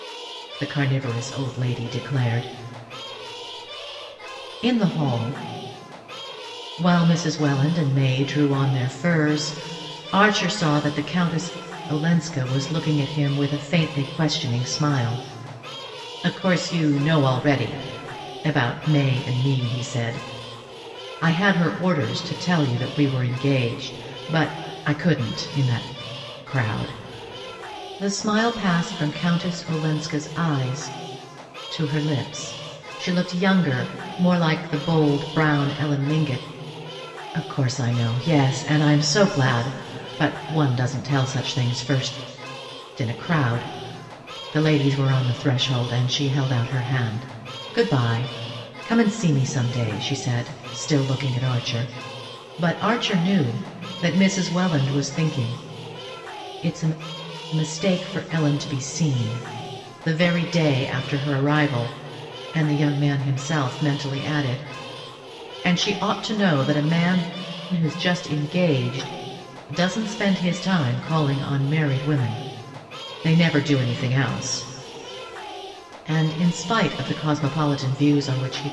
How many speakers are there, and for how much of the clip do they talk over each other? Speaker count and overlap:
one, no overlap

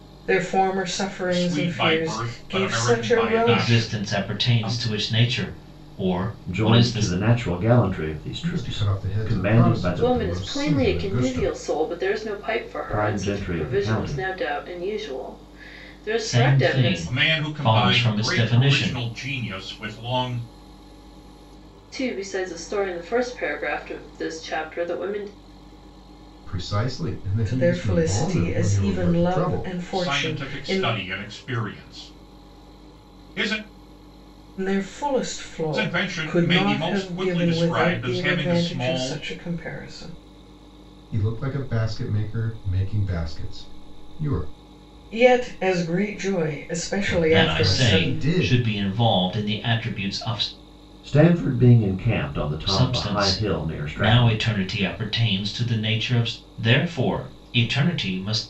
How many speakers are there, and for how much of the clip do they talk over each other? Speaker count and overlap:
six, about 37%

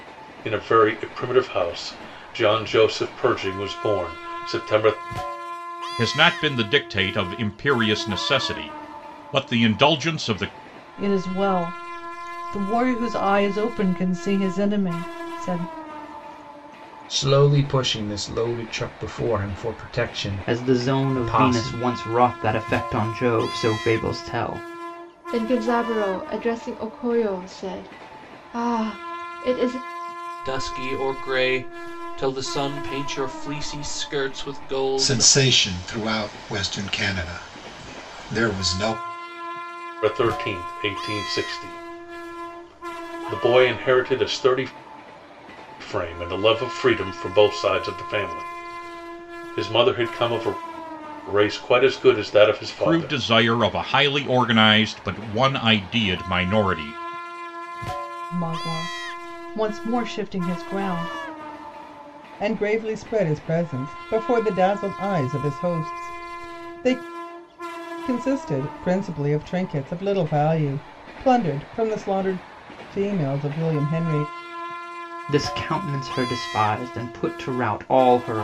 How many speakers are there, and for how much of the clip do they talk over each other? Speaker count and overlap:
eight, about 3%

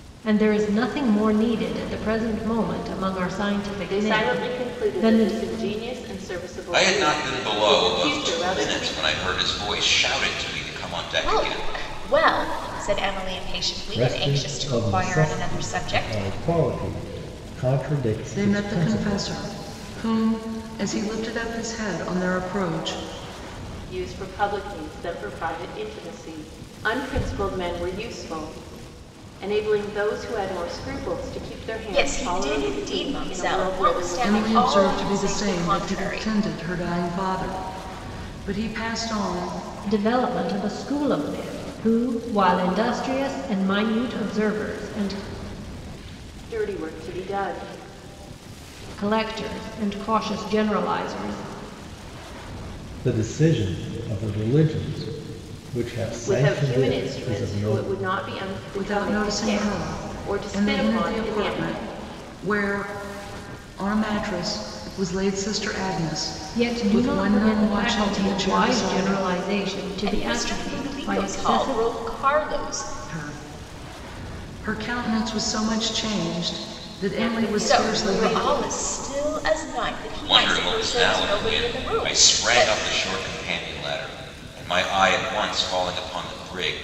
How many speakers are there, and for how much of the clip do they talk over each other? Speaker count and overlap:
six, about 29%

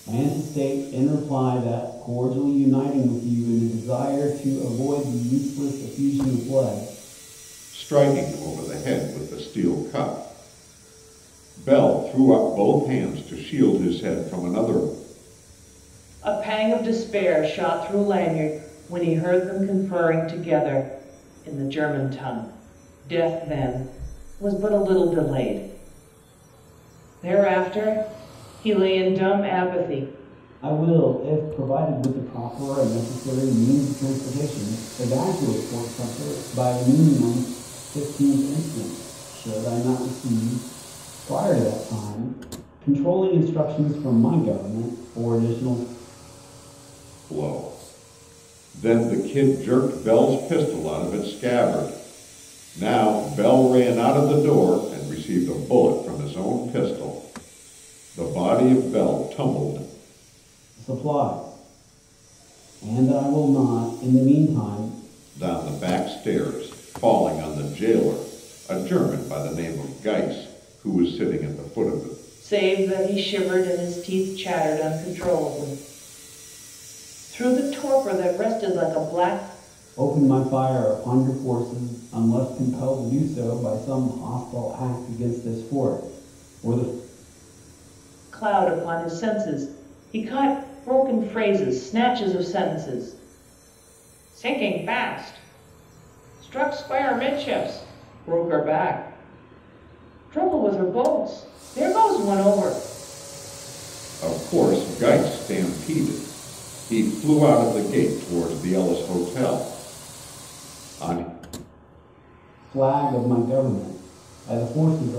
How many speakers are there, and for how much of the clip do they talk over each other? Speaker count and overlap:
three, no overlap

